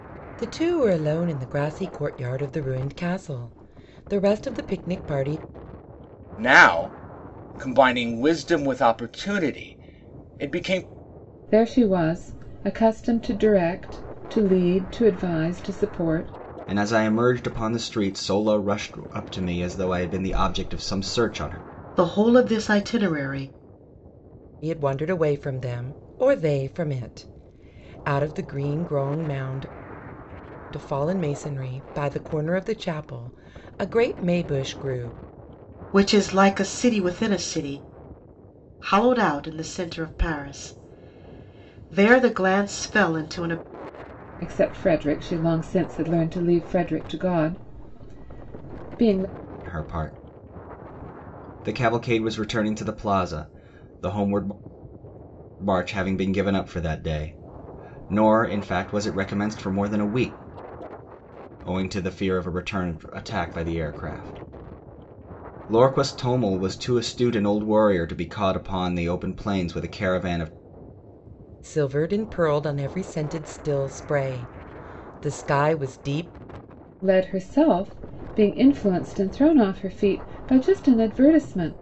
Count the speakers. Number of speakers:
5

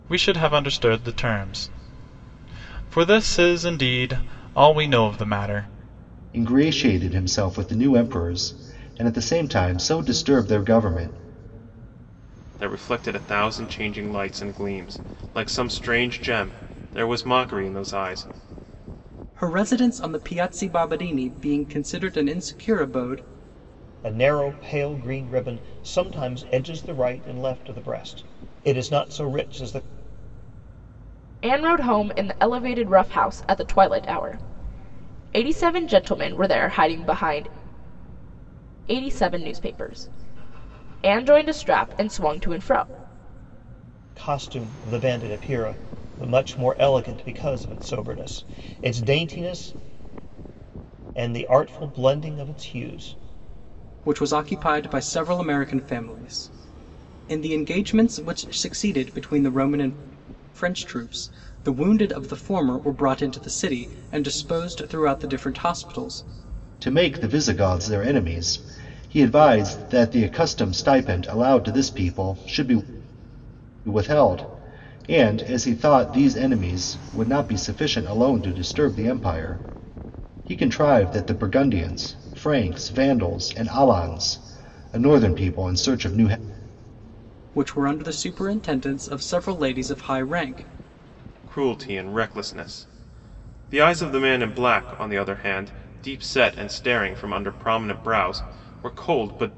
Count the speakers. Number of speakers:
6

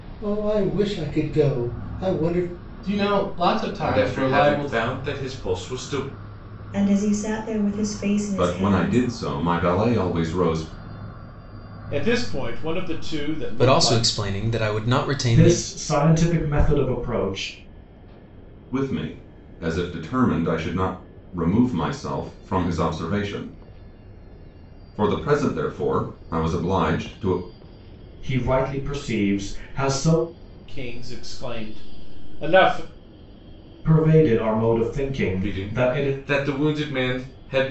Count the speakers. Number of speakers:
8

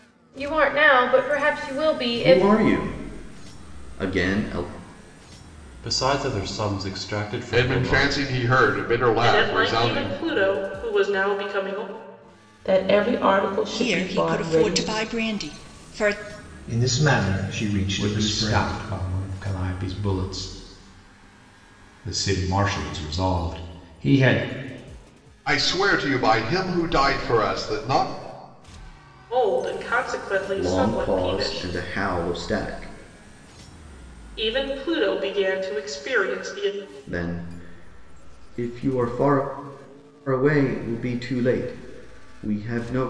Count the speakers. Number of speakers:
9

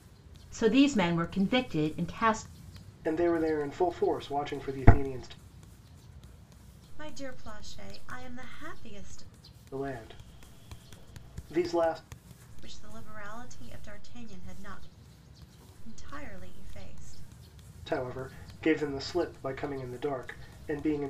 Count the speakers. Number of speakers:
3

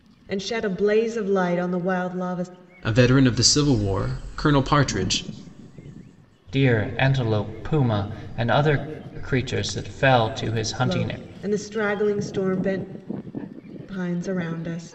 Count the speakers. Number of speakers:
3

